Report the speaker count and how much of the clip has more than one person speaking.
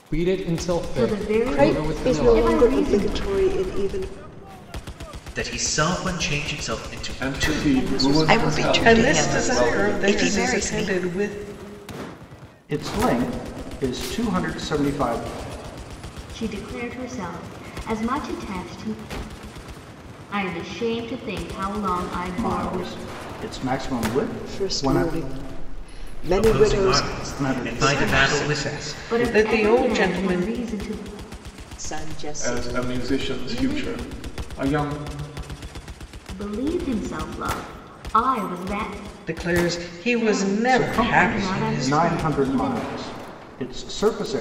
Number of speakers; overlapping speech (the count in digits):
9, about 36%